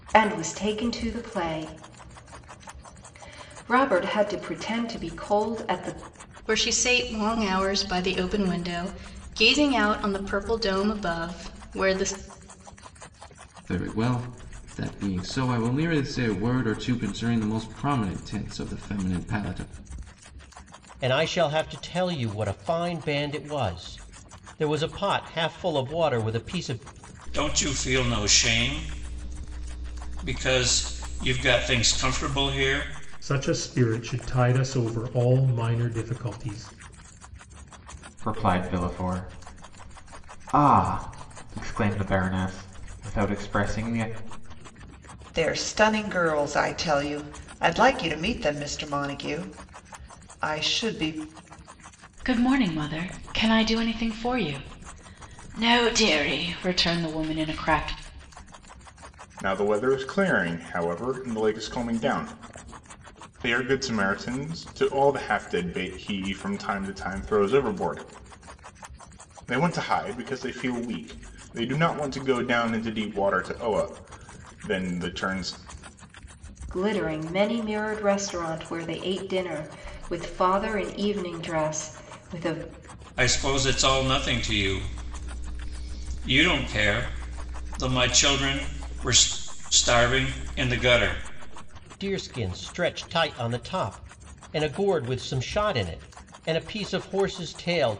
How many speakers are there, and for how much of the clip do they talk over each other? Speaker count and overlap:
ten, no overlap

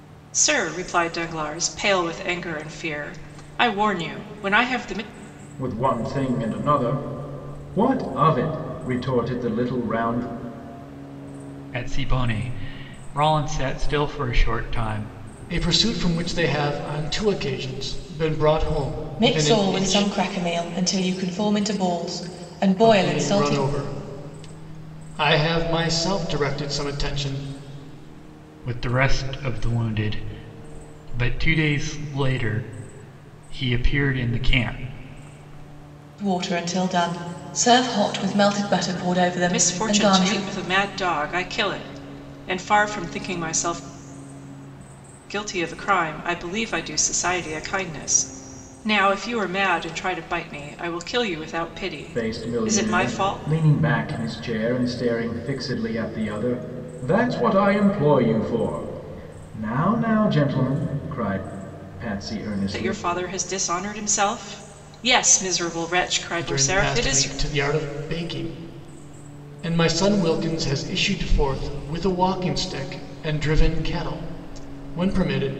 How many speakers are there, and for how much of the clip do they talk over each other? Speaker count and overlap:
five, about 7%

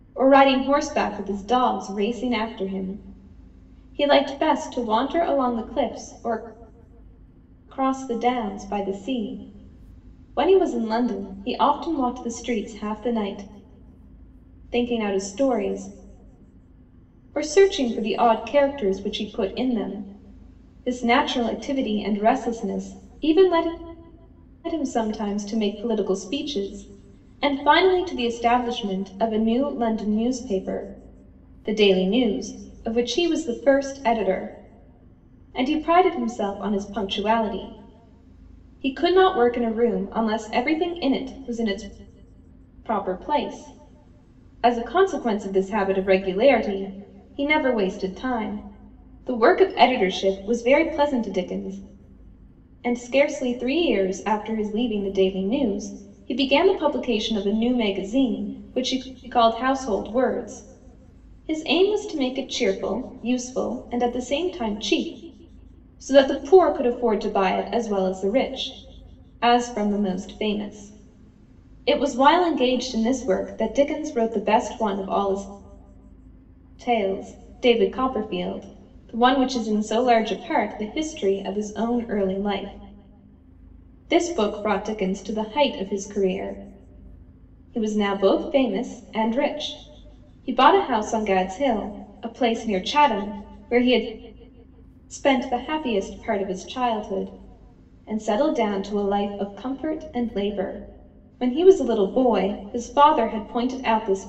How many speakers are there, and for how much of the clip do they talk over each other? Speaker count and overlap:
one, no overlap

